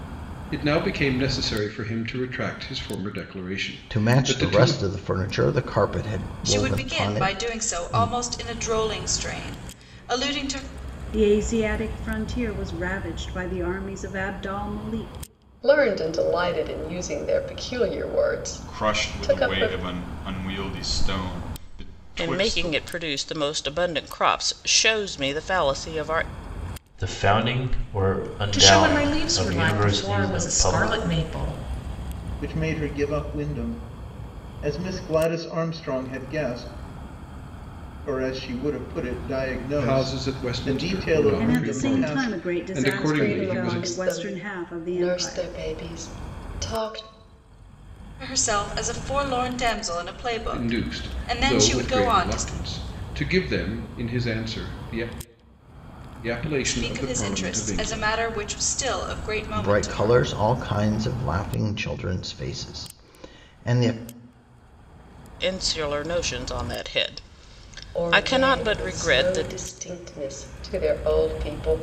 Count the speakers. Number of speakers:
ten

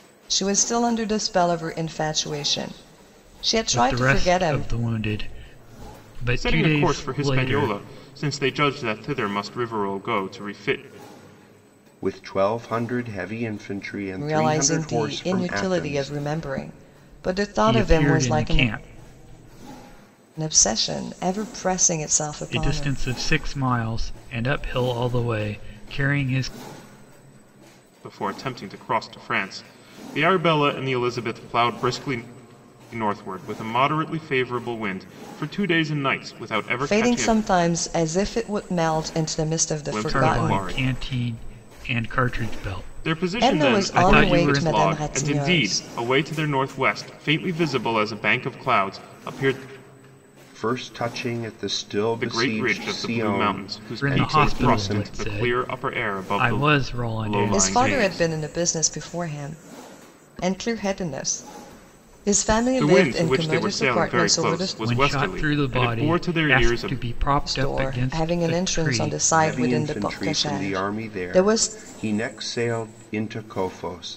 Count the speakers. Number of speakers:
four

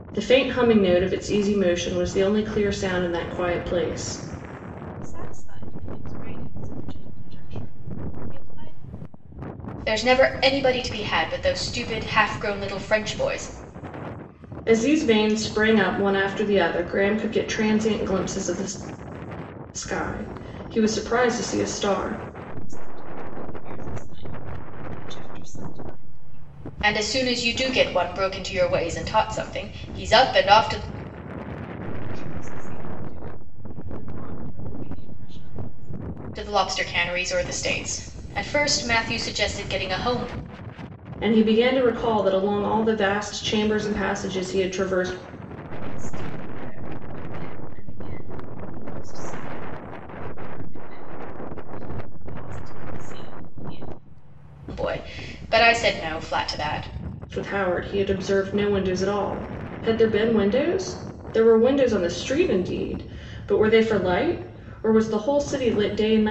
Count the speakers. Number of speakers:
three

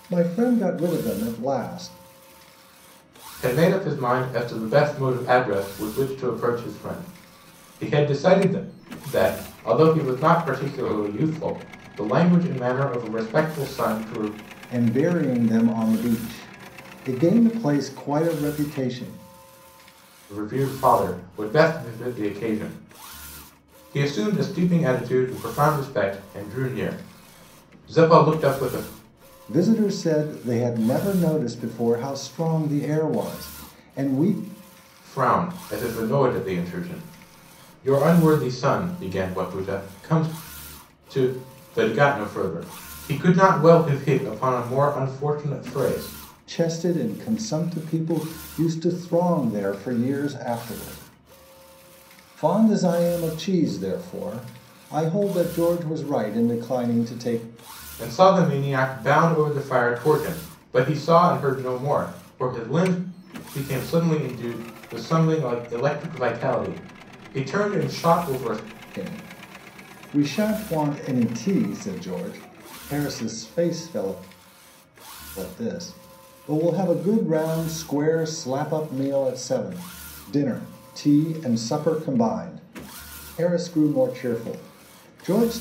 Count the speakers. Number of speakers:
two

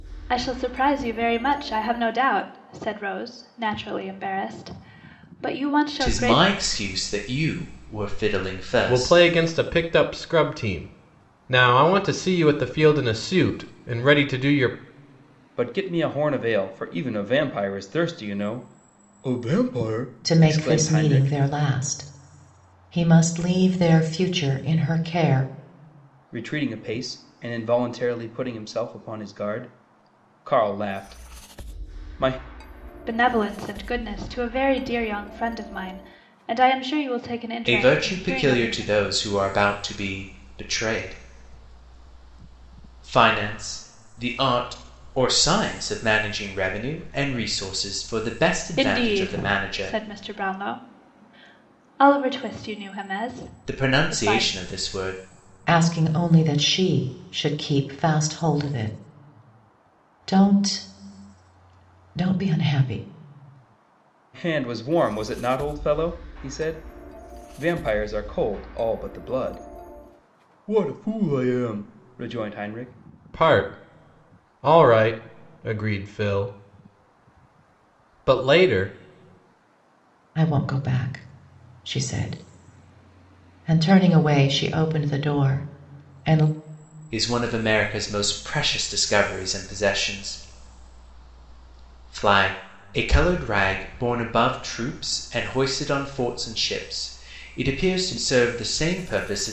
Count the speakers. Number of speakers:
five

